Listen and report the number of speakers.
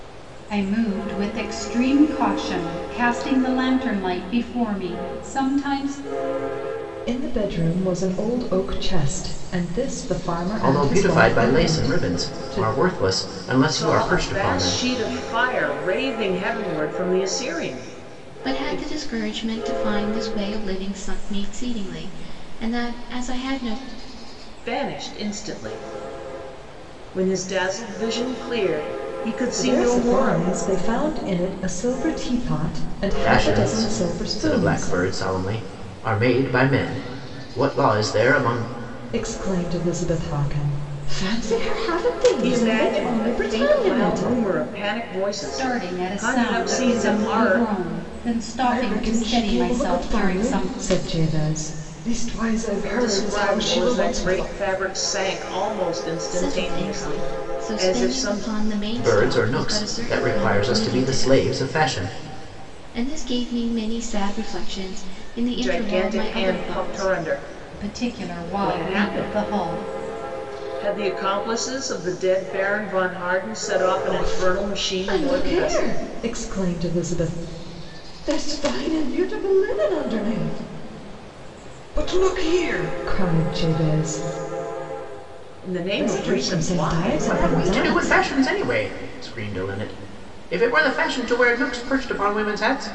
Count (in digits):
5